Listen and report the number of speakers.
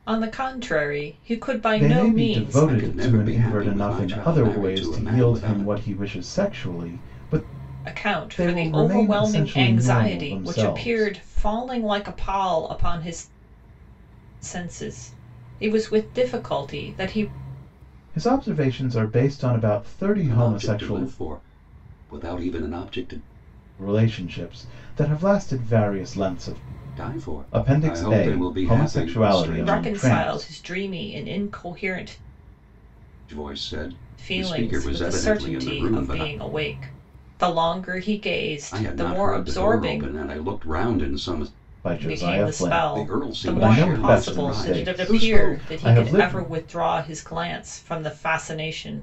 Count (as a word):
three